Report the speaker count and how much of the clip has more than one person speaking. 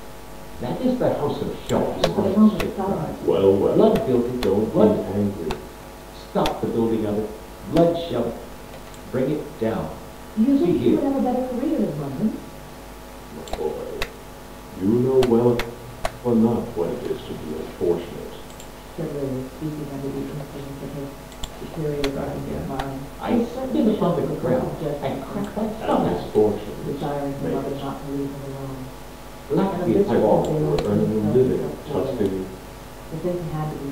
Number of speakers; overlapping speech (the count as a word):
three, about 36%